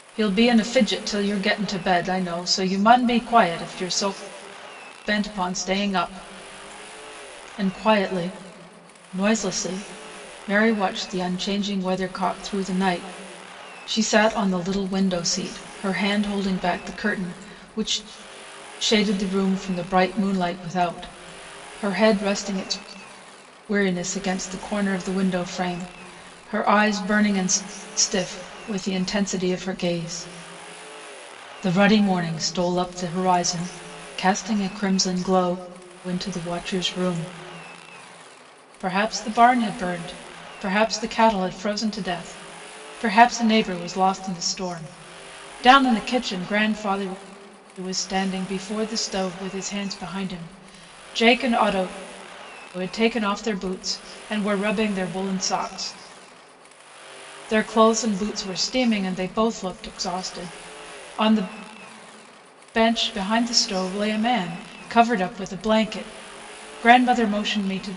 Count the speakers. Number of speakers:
one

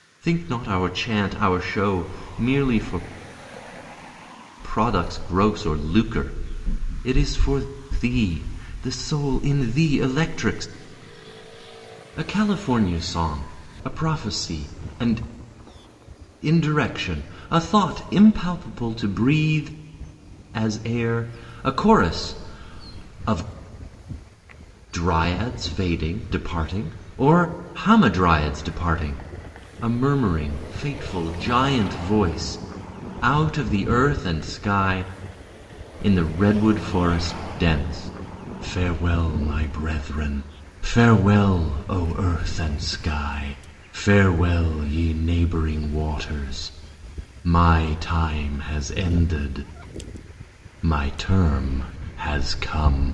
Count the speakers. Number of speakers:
one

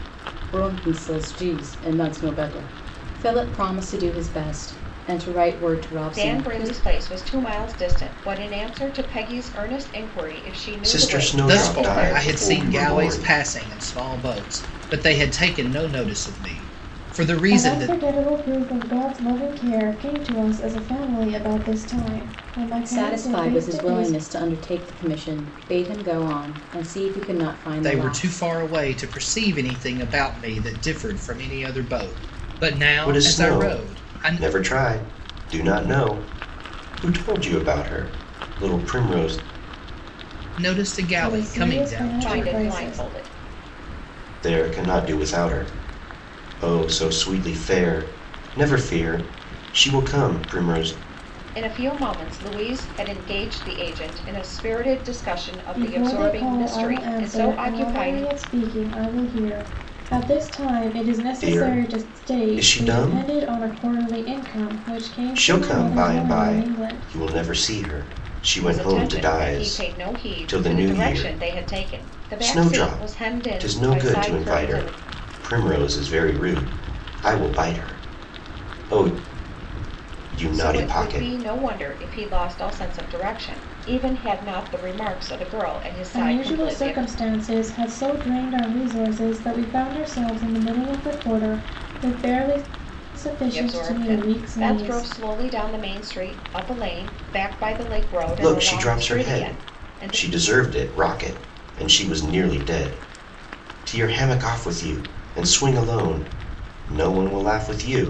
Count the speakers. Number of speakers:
five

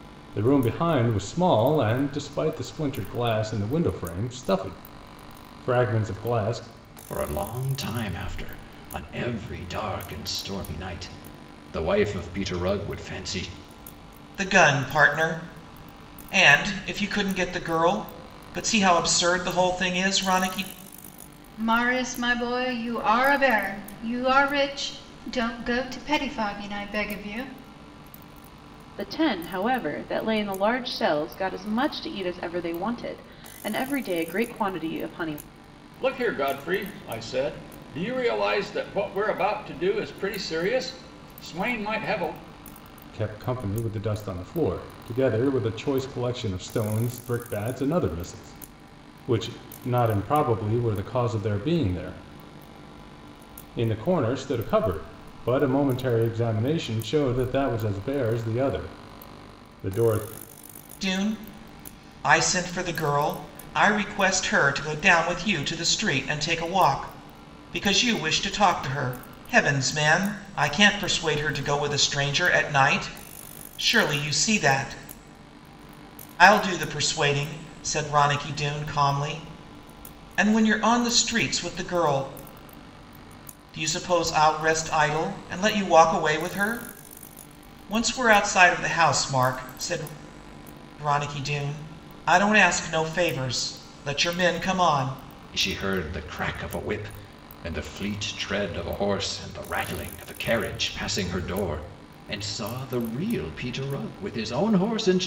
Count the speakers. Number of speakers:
six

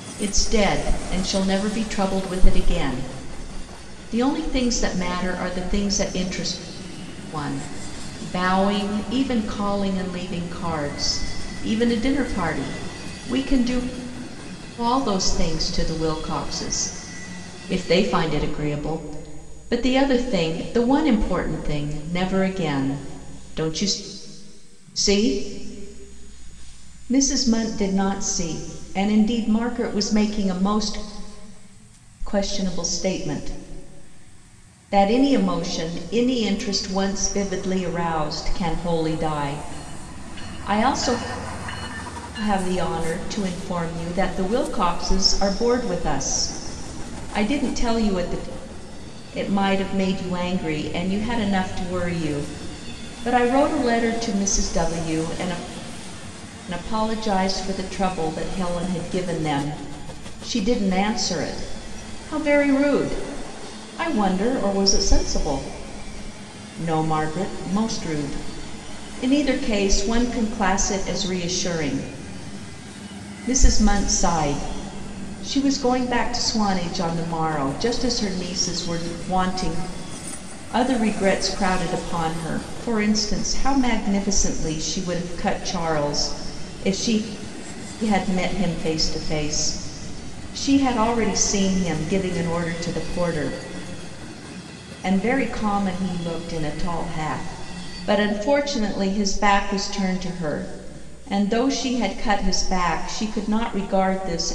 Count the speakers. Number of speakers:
one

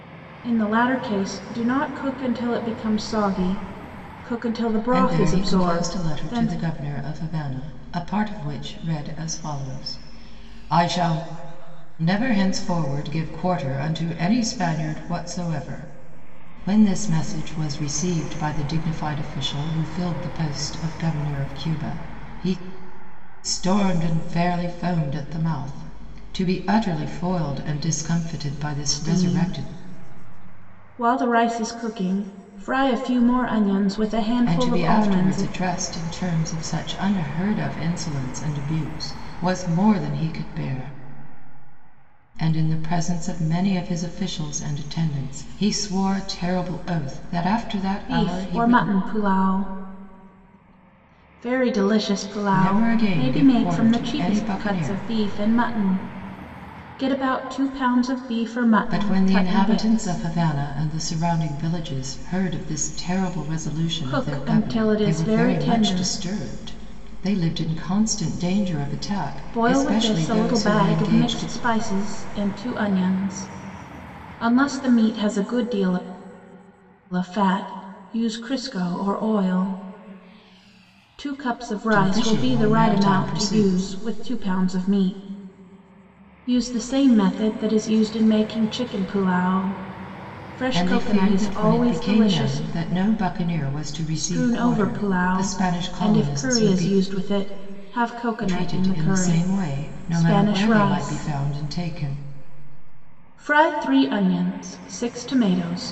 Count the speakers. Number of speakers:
two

